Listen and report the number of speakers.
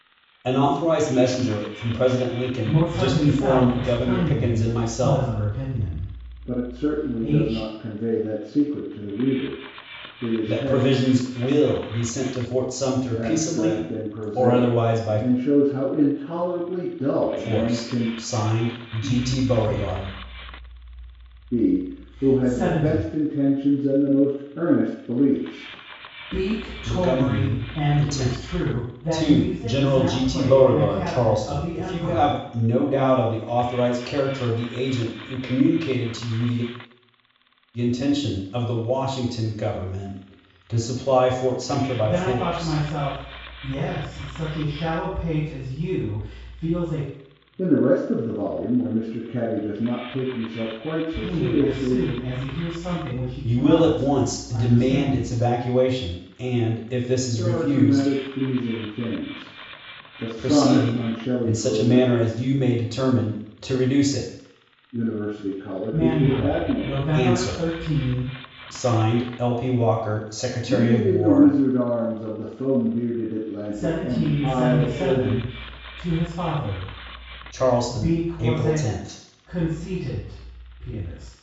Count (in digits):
3